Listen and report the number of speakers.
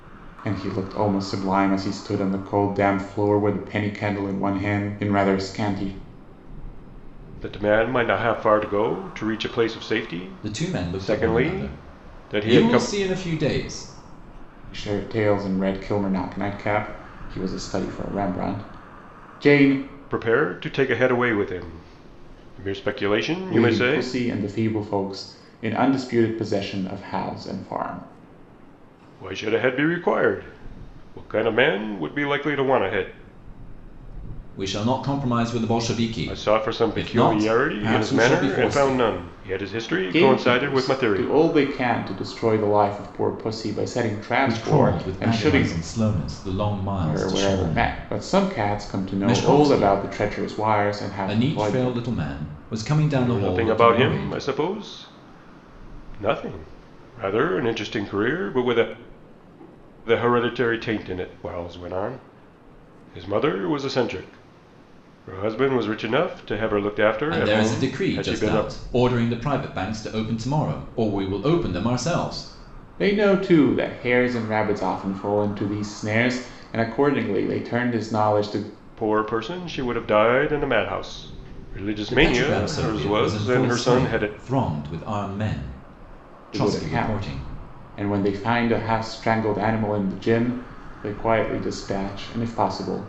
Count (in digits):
3